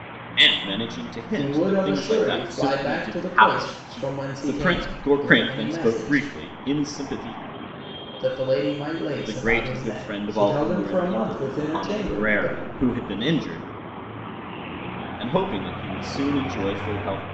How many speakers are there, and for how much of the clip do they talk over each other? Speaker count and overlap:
2, about 48%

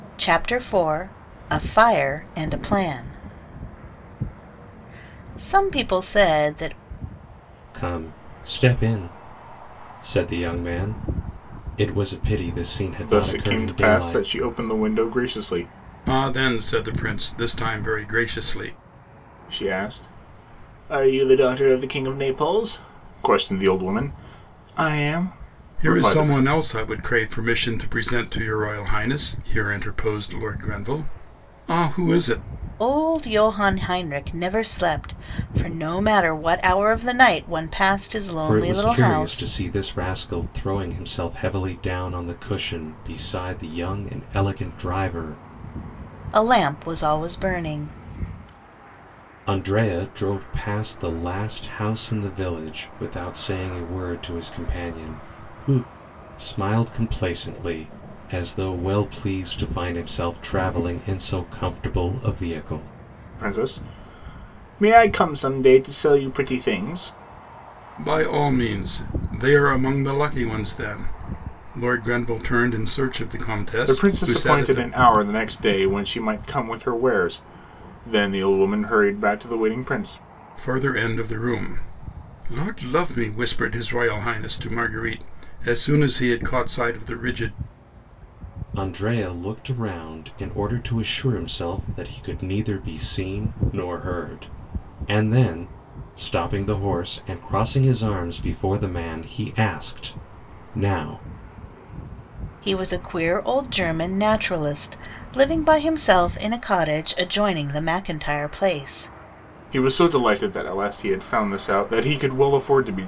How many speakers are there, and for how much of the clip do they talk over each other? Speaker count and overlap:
4, about 4%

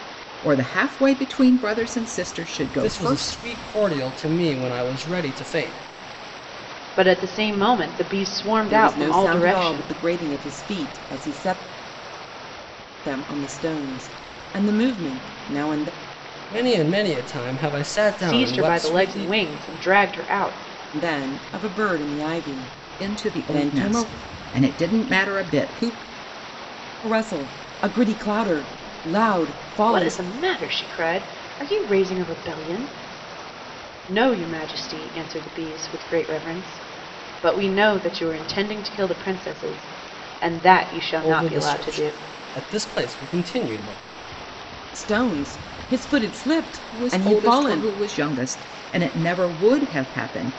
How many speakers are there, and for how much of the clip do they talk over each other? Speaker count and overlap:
4, about 13%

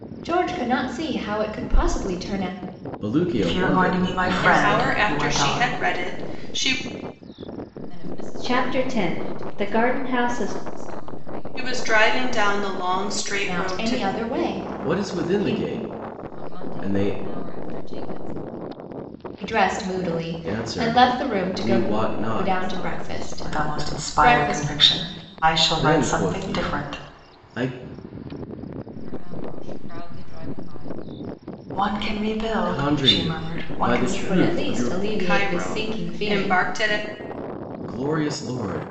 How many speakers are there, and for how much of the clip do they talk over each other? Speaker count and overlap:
6, about 45%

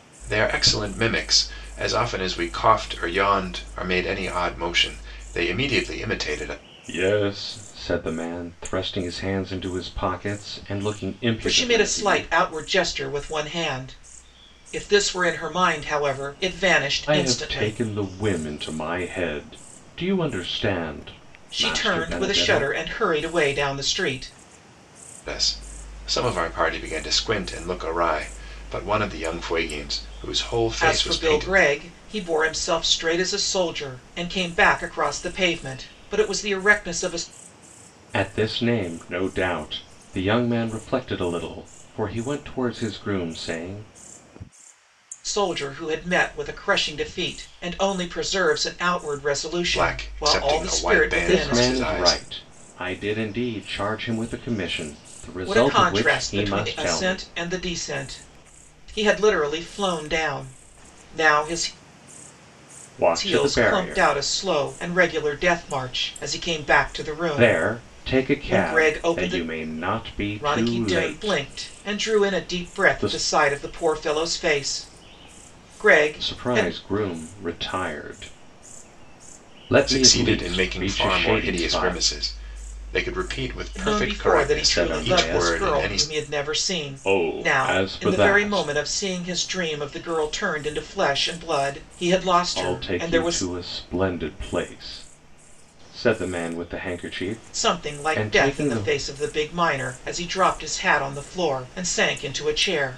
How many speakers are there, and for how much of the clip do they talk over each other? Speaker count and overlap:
3, about 23%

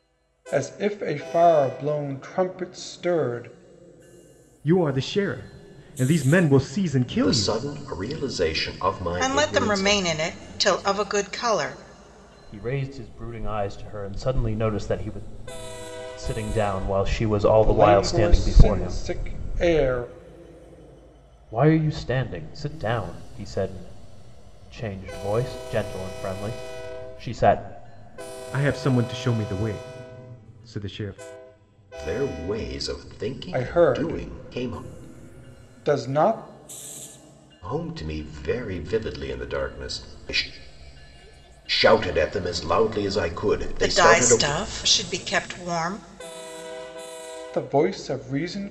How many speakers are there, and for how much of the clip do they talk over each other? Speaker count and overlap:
5, about 10%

